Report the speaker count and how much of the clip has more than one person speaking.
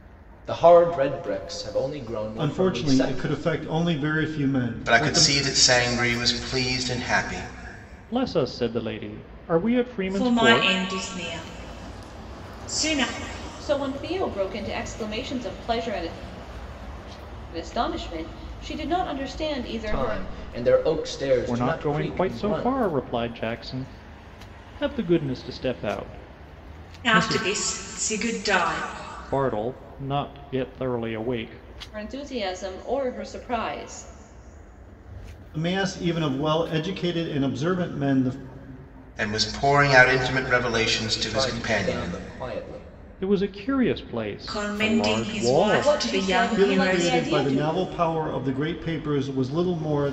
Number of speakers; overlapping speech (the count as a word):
six, about 19%